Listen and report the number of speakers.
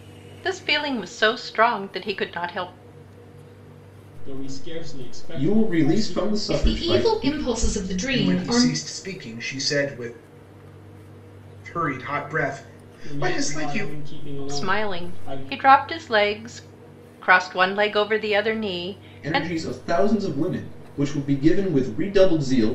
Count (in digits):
5